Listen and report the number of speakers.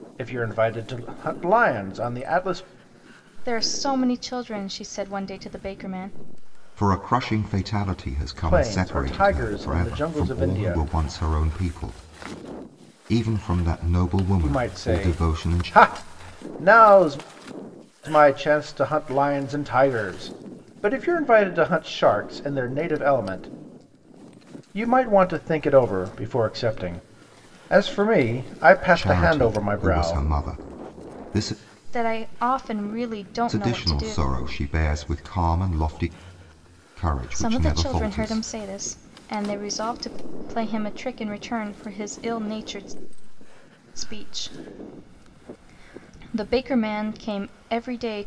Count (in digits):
3